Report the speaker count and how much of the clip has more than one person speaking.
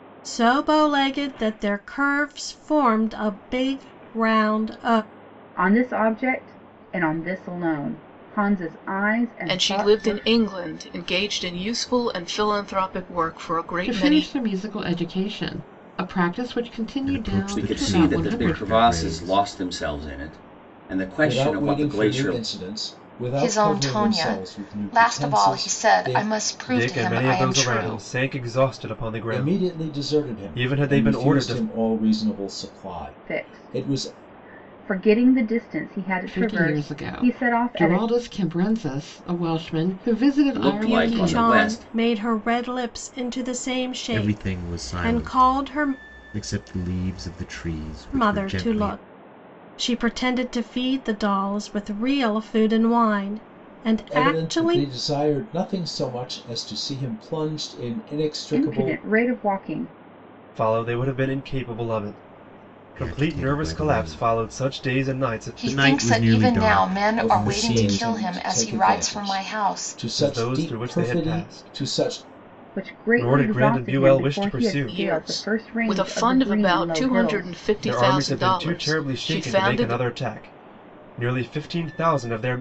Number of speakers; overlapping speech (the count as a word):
nine, about 44%